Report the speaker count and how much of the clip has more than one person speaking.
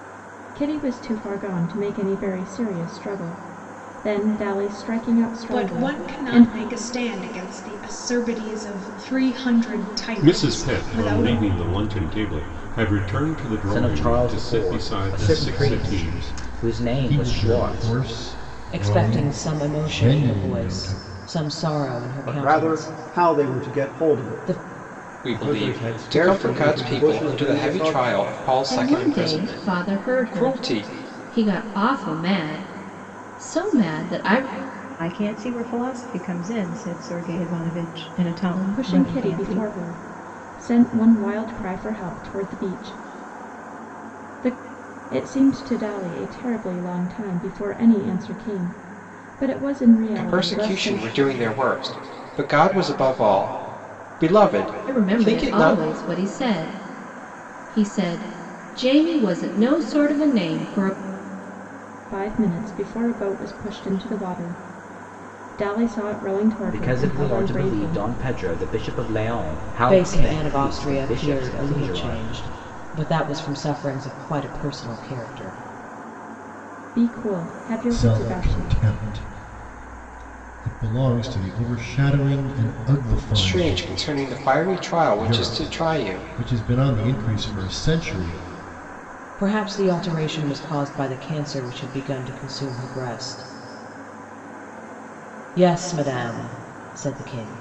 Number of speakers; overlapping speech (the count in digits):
10, about 27%